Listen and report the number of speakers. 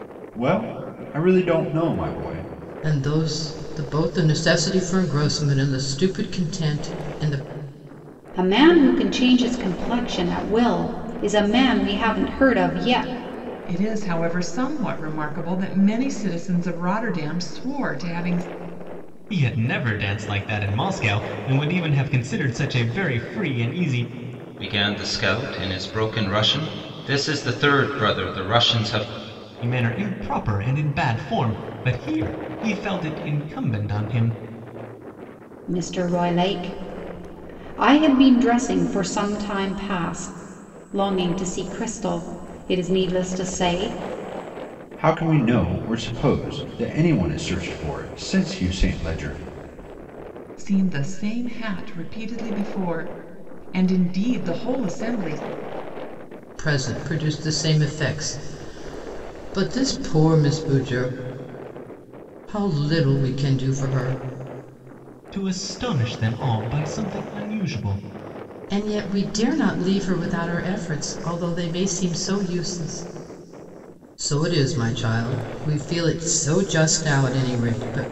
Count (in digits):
6